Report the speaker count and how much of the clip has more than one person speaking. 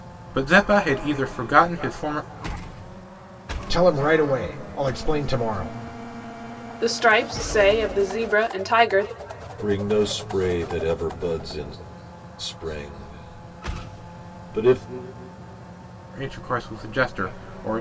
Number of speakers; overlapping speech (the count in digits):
4, no overlap